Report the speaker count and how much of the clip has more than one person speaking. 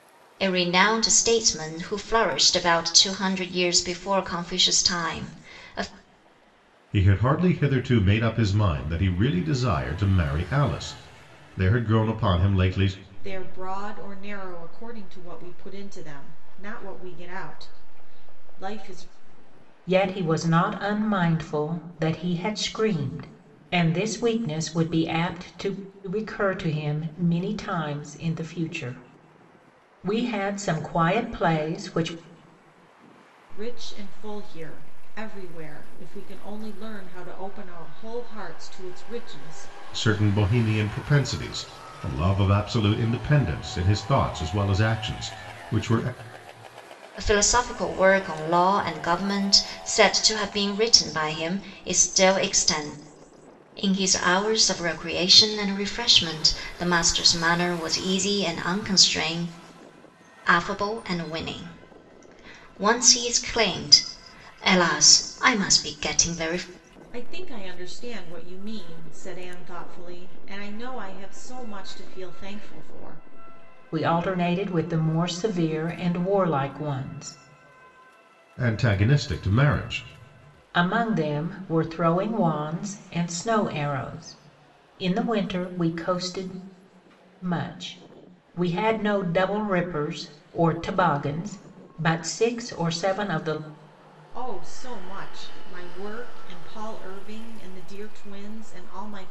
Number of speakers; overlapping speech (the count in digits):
4, no overlap